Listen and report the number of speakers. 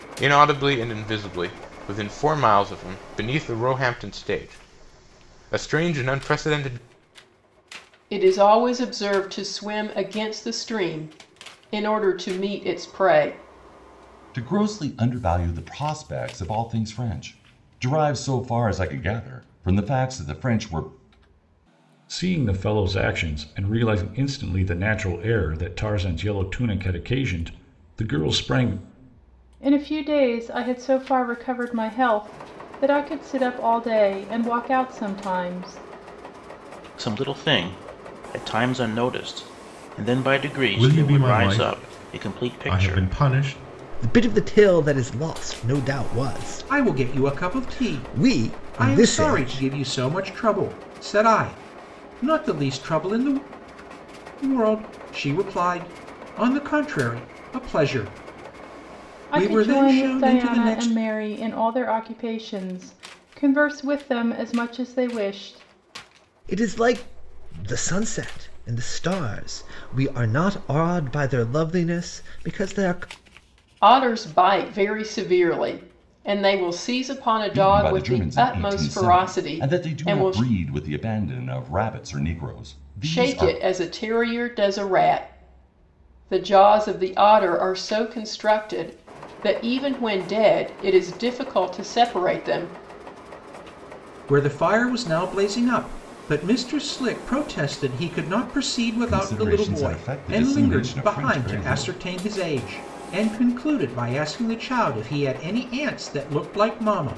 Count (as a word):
nine